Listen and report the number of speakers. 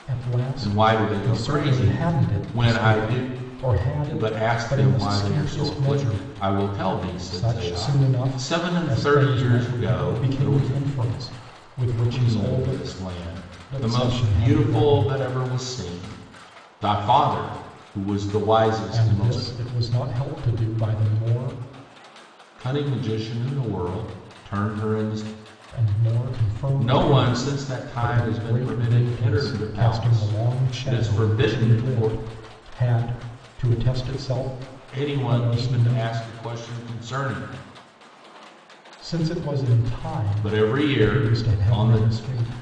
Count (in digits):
2